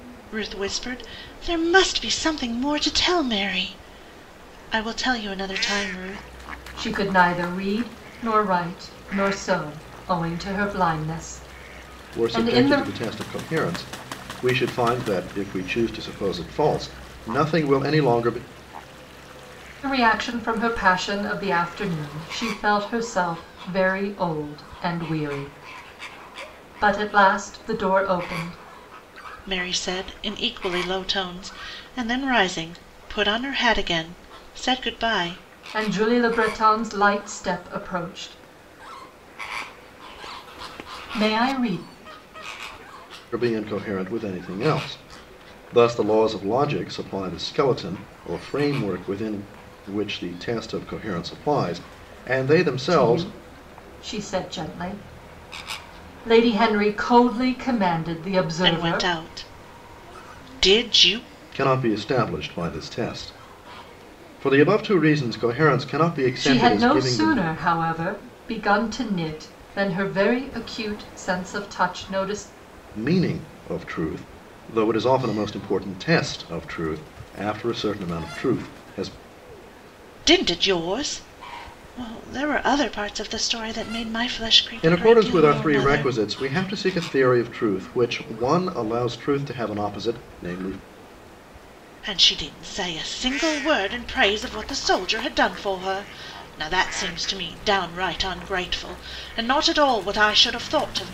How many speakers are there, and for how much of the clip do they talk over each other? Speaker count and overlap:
3, about 4%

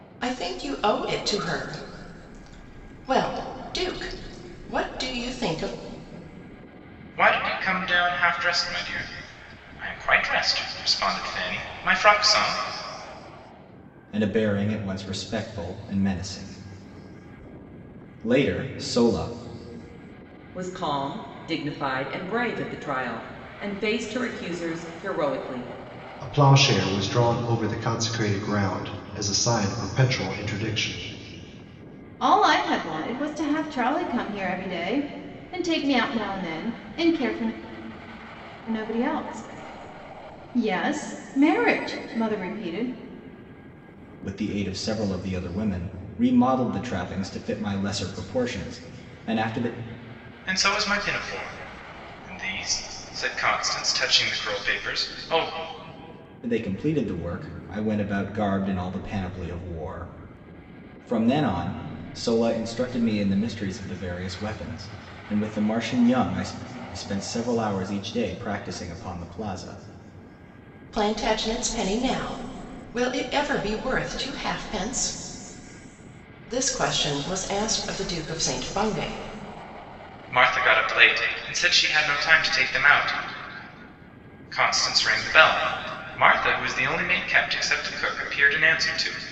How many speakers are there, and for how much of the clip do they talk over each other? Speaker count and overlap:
6, no overlap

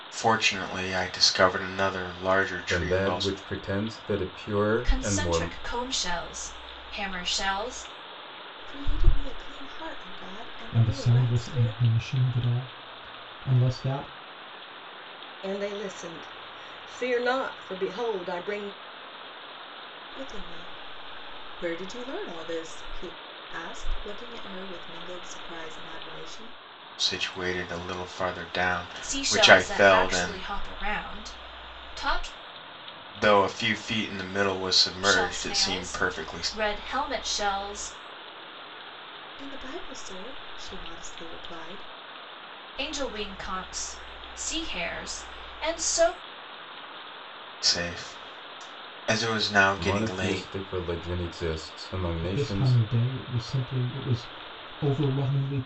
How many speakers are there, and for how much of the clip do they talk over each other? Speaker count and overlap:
6, about 13%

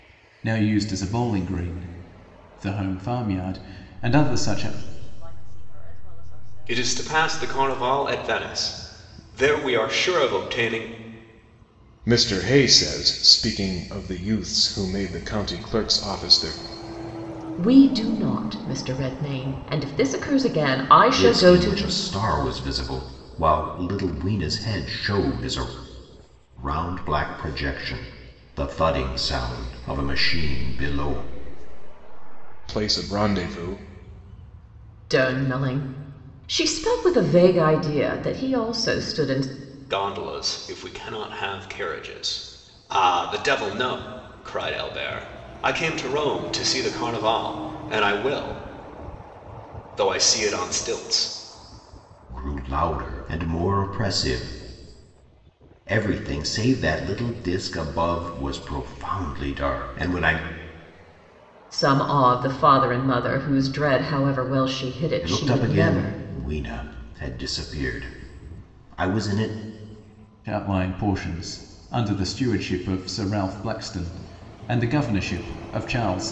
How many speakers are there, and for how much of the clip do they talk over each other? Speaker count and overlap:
6, about 5%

